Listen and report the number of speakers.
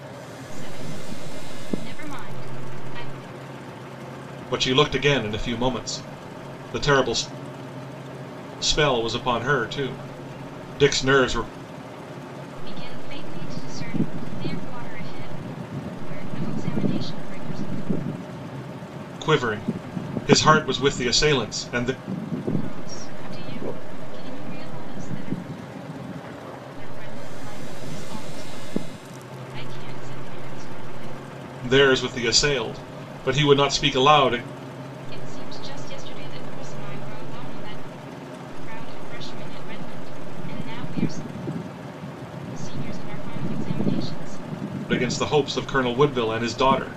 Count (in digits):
2